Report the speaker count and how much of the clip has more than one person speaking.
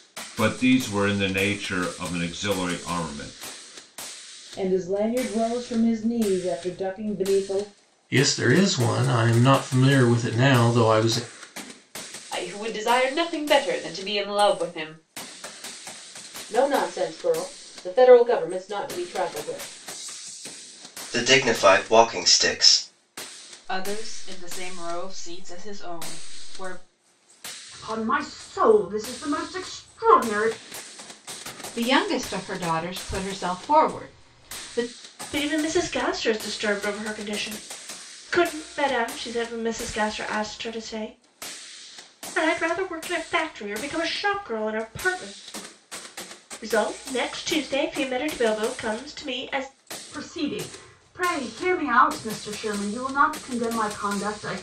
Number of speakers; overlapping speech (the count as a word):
ten, no overlap